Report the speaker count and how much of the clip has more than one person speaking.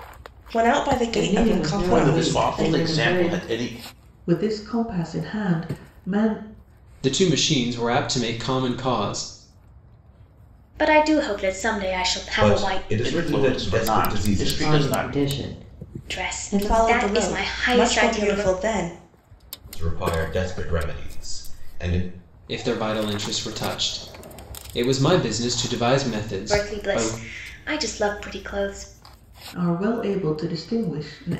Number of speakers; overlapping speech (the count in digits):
7, about 26%